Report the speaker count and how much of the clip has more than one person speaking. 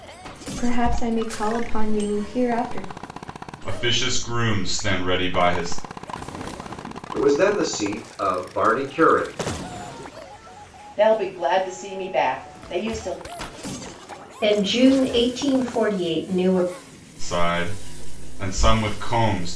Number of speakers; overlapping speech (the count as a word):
five, no overlap